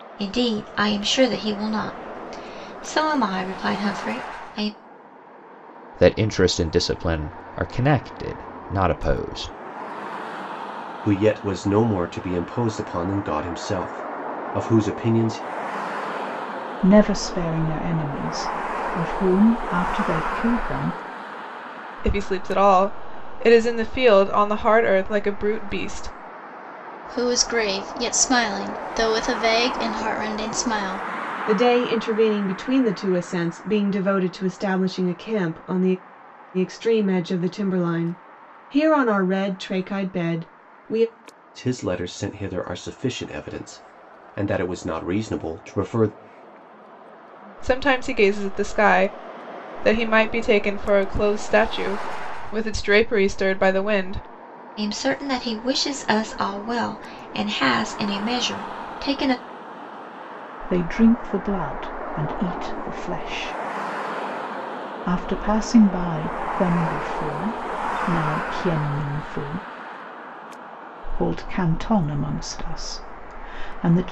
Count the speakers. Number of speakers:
seven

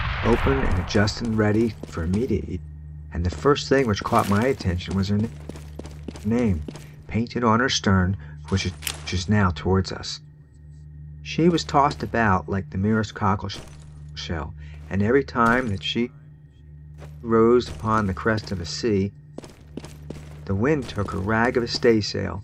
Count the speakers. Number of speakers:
one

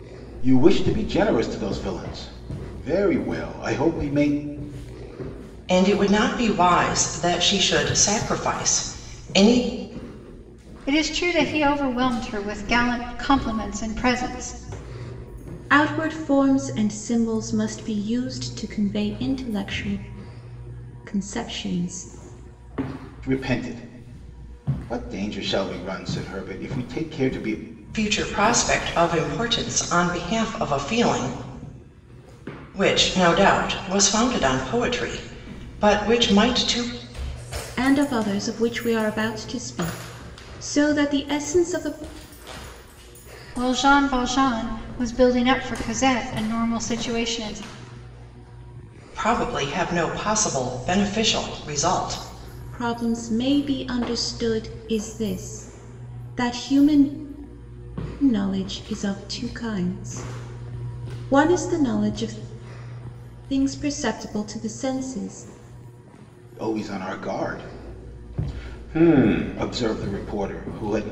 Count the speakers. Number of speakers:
four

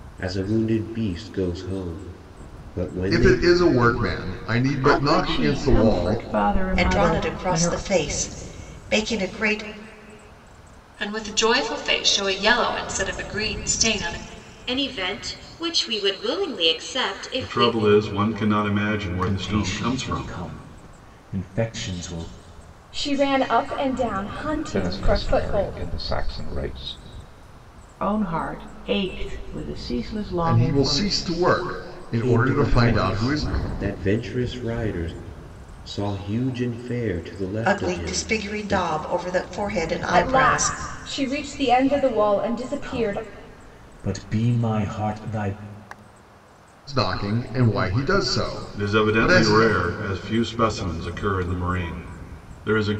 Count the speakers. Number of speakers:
ten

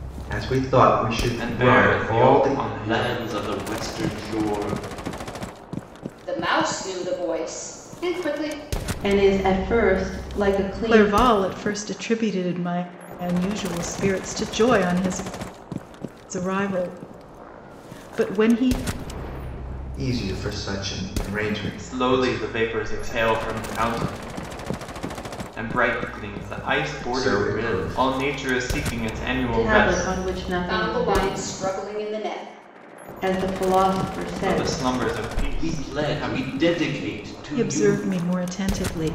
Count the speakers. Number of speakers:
six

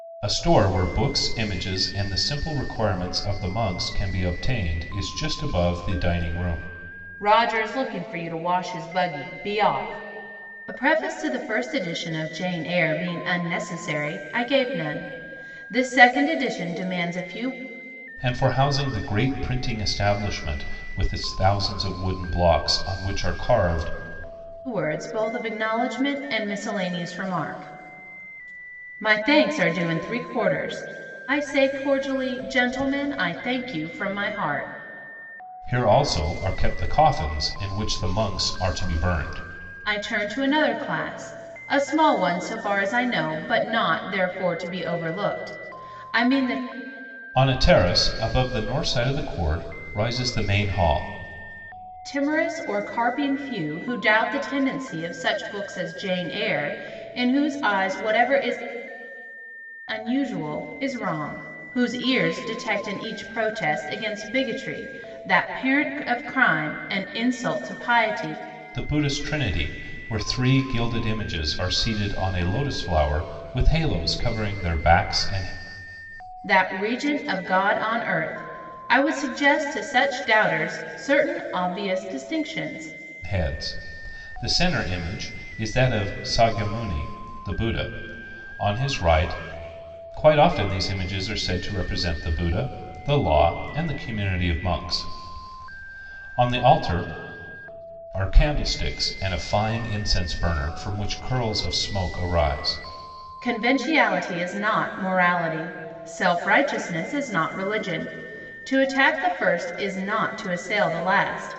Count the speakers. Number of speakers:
two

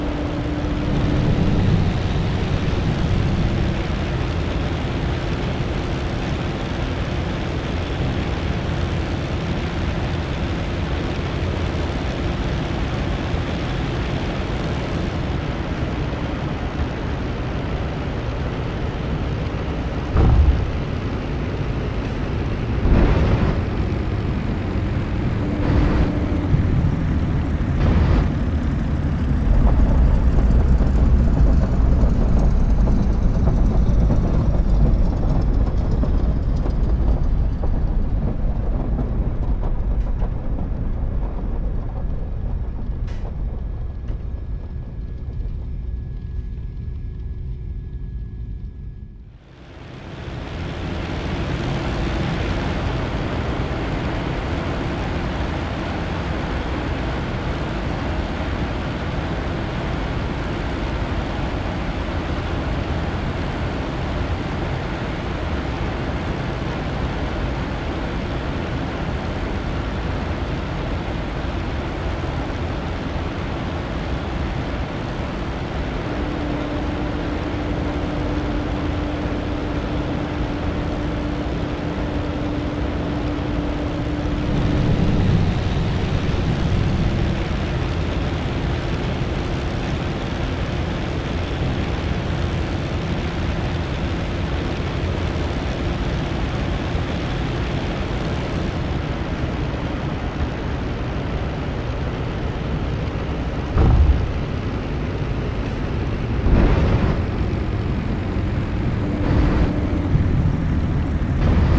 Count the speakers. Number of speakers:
zero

